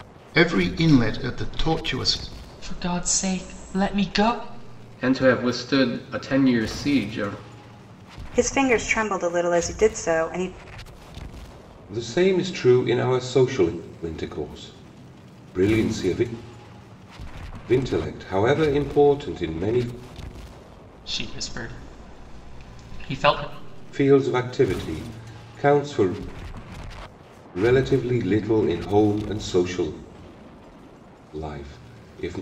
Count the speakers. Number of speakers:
five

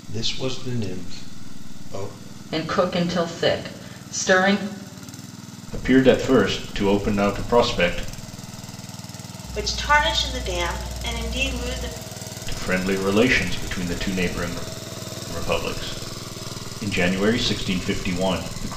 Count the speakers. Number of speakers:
four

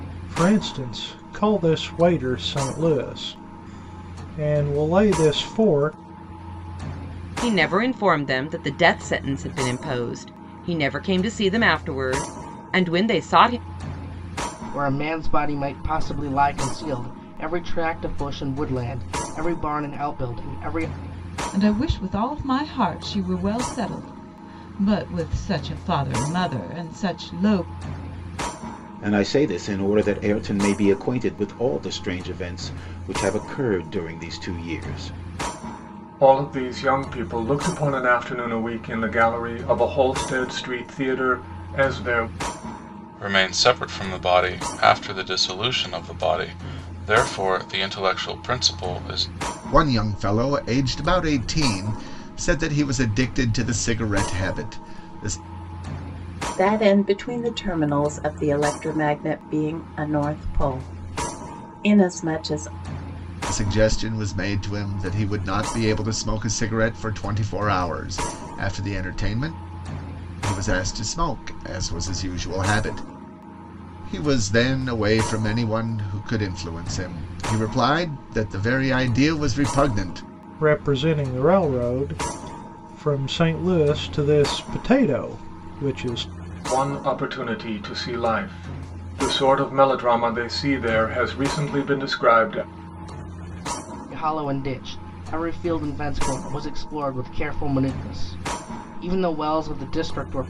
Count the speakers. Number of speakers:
nine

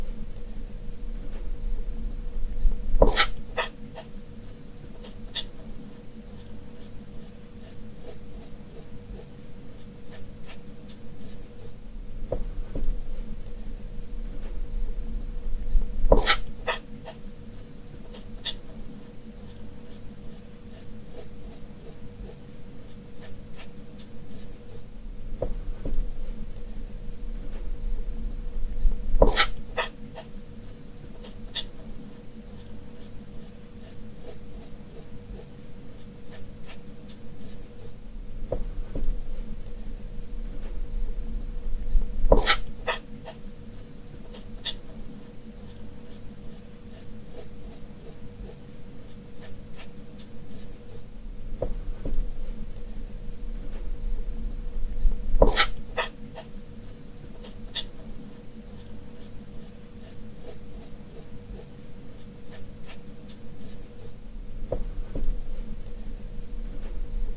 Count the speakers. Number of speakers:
zero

